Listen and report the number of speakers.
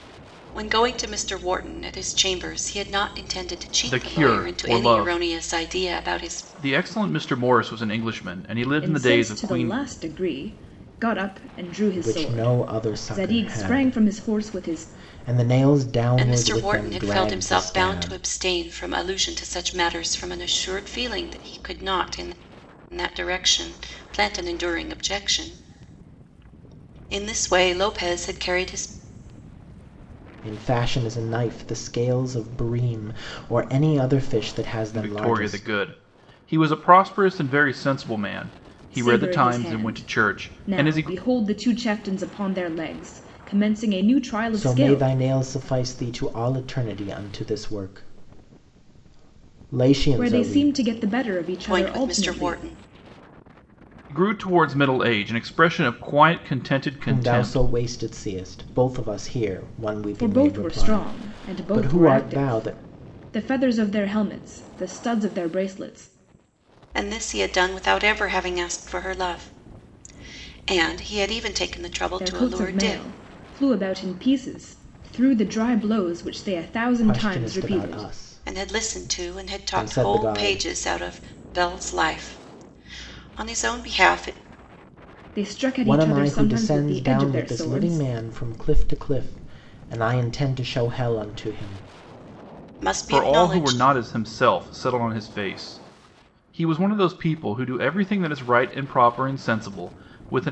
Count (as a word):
four